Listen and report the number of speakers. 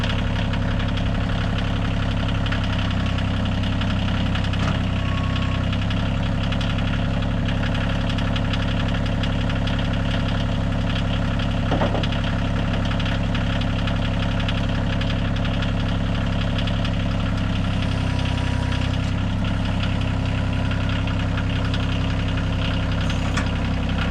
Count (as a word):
zero